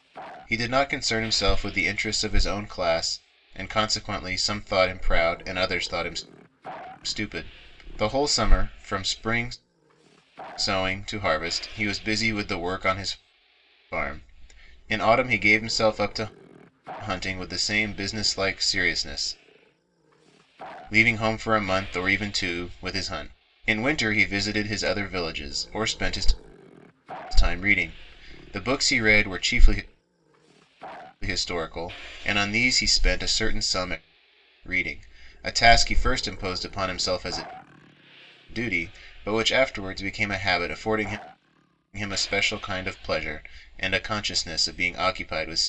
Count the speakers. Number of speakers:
1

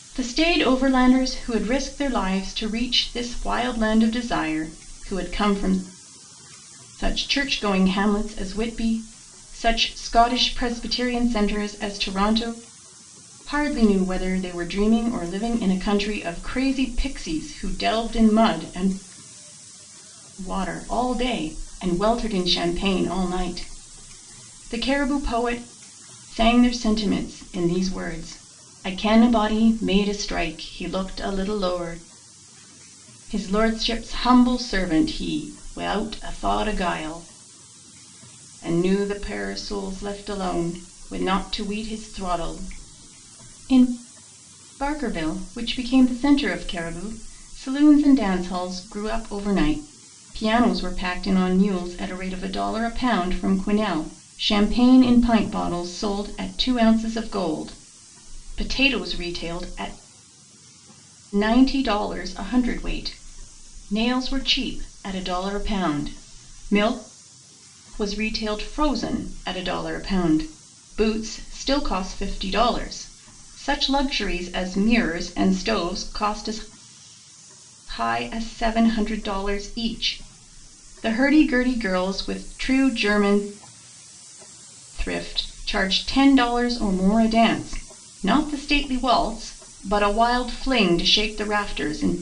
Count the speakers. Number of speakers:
1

